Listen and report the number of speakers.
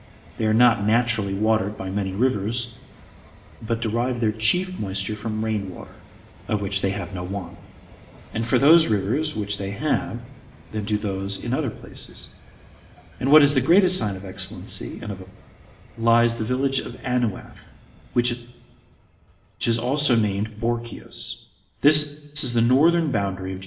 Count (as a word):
one